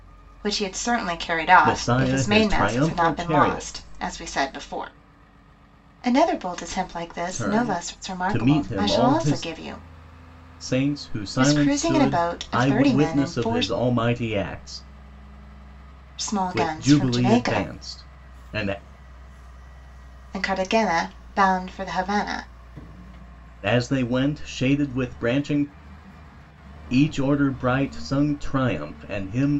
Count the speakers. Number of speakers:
two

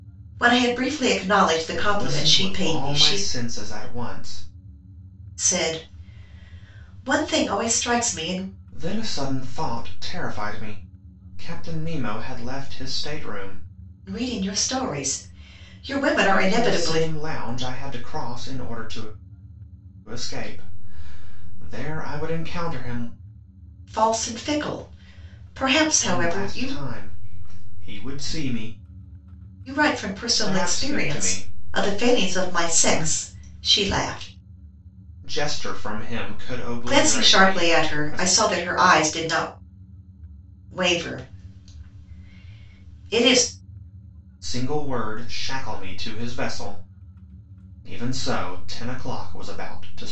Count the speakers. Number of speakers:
two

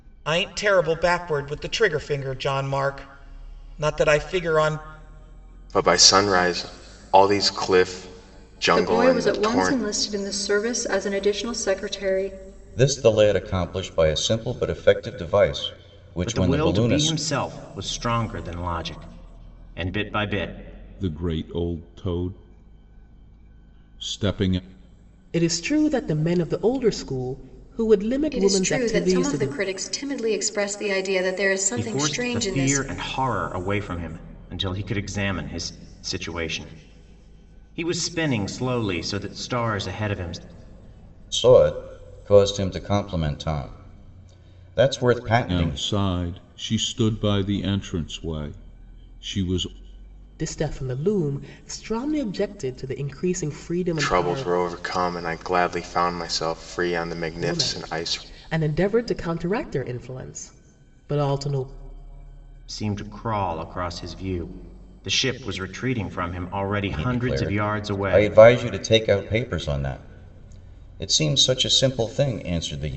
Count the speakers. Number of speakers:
eight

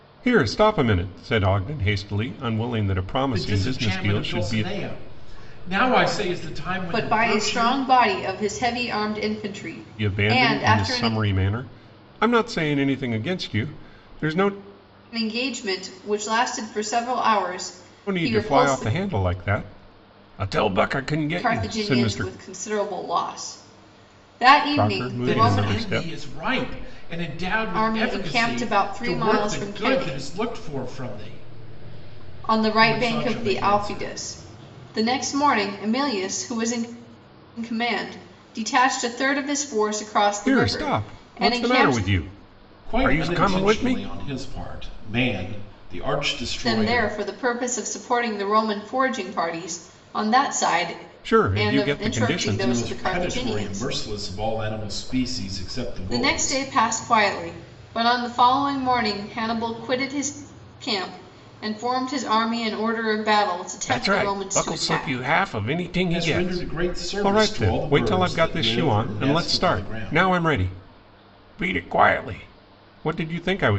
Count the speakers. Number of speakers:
three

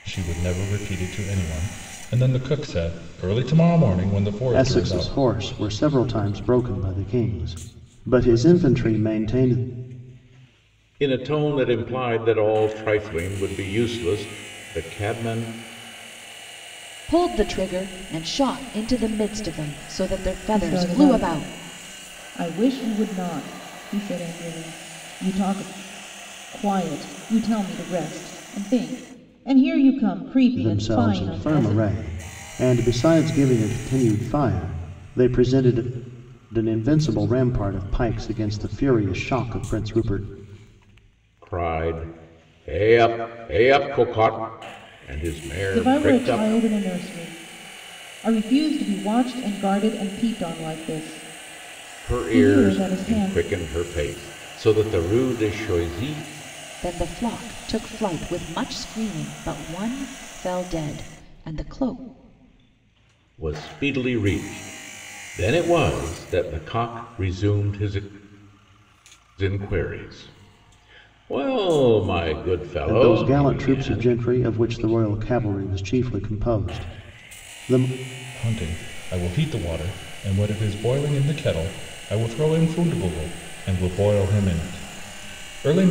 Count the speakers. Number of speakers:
five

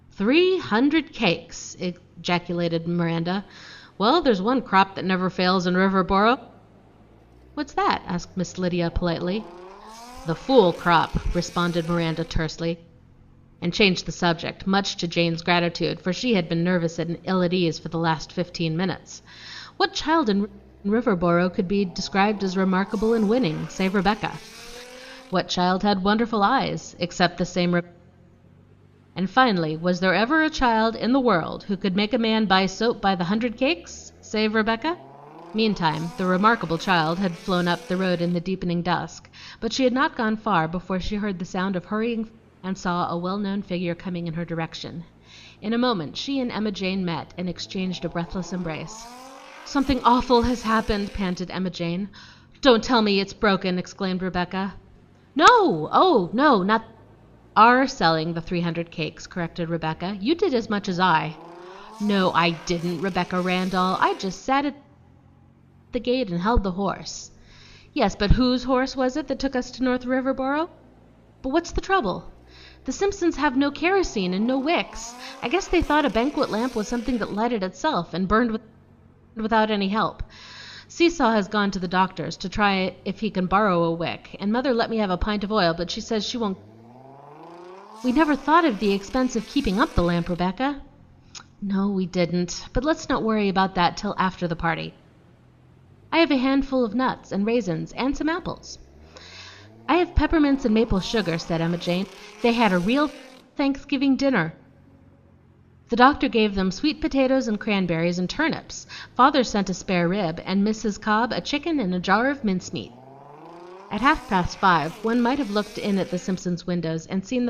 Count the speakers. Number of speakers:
one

